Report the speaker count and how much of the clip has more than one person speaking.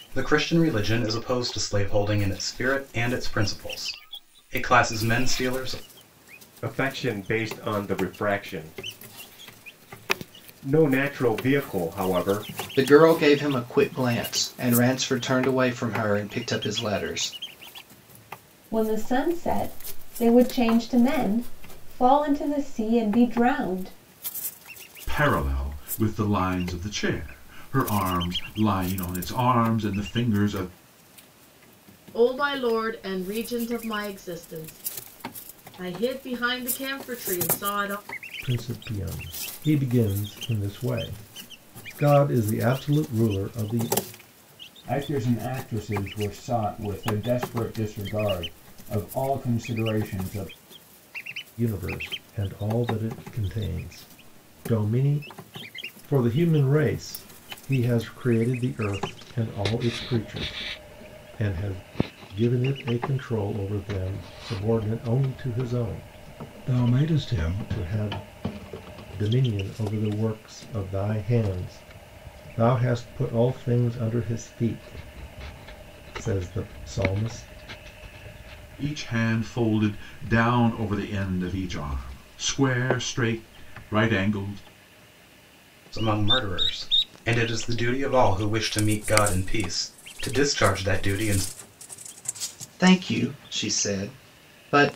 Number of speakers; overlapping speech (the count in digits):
8, no overlap